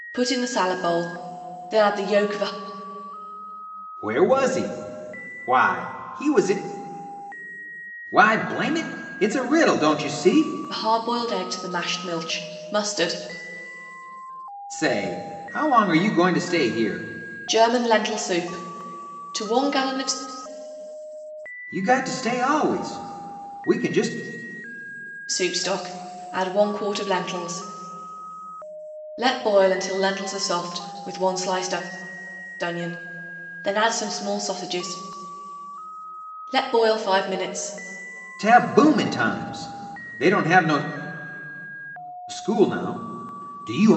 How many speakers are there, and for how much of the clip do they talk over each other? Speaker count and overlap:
2, no overlap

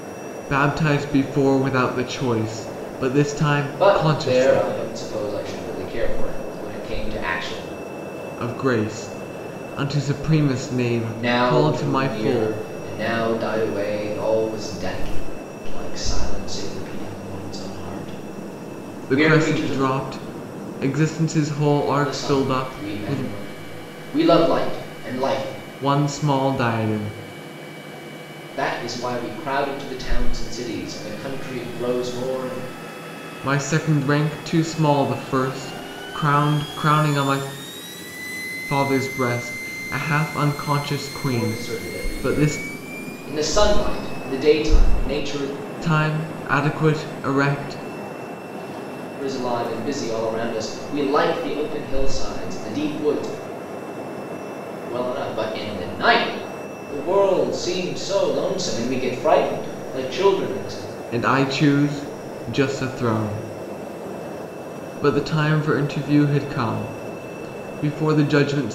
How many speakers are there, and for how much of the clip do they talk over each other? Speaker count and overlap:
2, about 9%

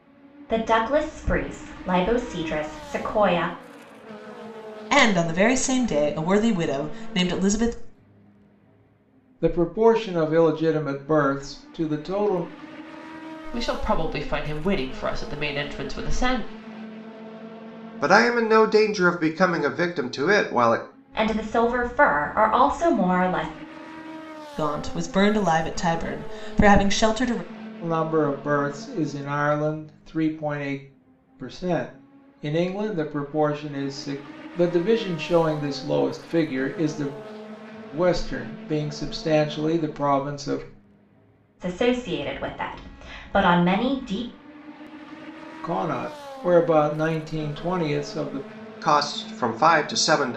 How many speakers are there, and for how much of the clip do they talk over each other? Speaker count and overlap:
5, no overlap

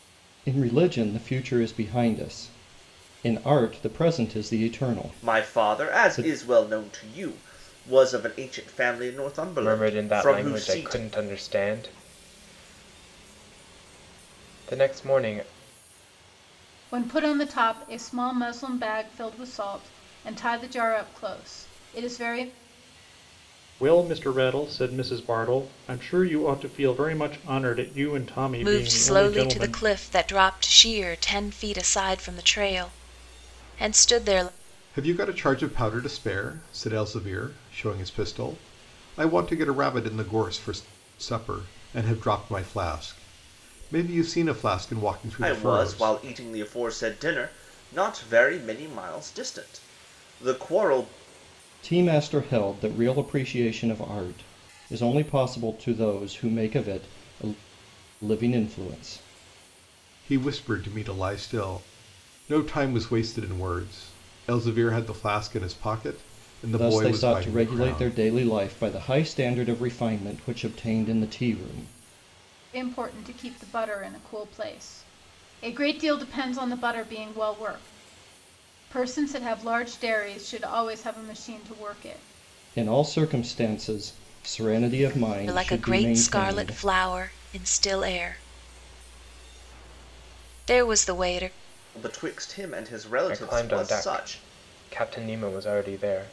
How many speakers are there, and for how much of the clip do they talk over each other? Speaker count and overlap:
7, about 9%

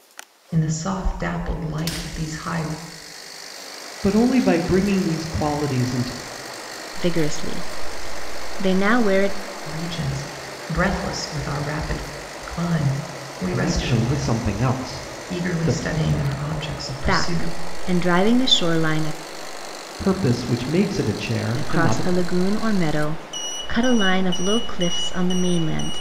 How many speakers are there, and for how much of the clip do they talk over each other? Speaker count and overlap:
3, about 10%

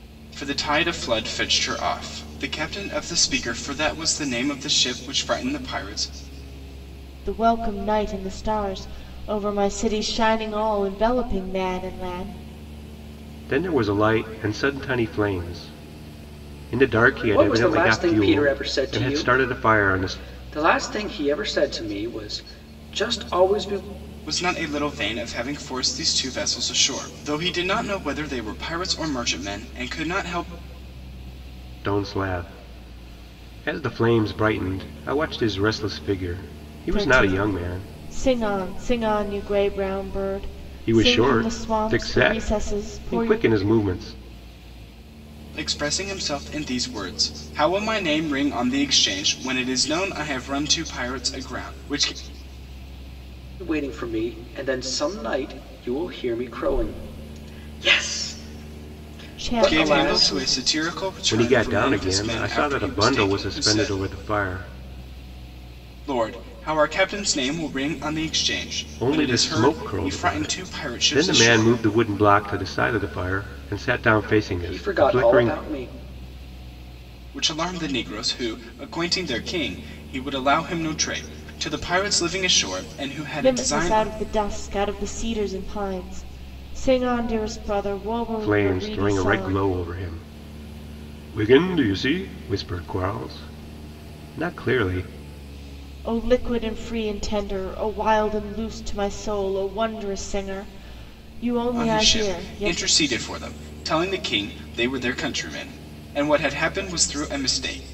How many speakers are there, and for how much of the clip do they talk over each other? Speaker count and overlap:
4, about 16%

